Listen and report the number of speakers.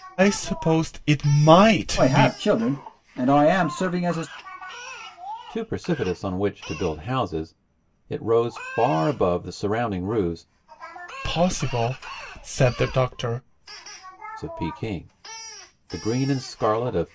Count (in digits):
3